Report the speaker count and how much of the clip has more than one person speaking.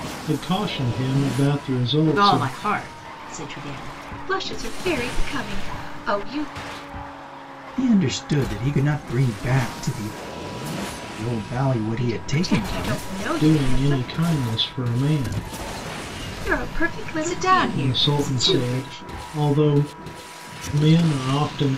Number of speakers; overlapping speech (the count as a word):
four, about 20%